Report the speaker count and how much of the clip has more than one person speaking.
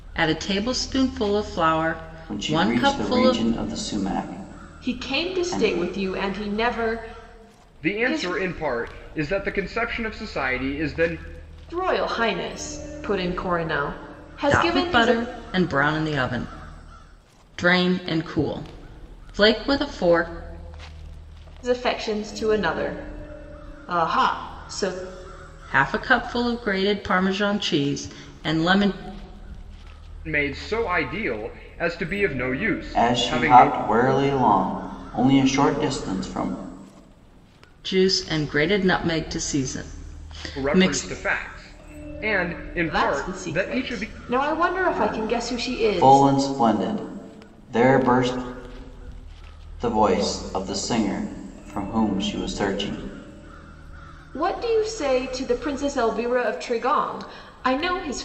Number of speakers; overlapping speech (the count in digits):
4, about 13%